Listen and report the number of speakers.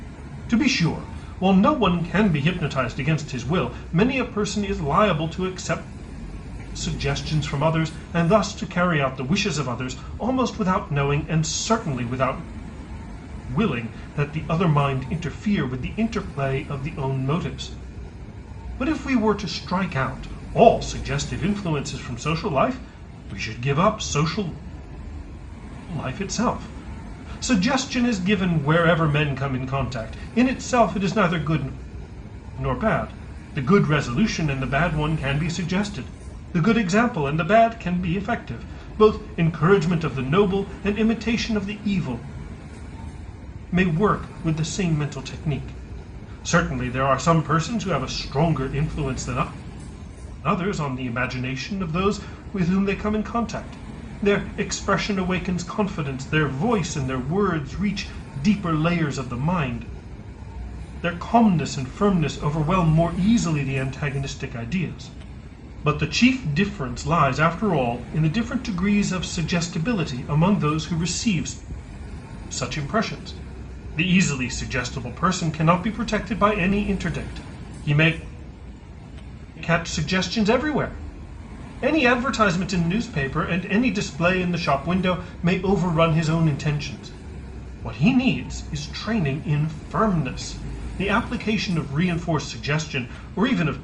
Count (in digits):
1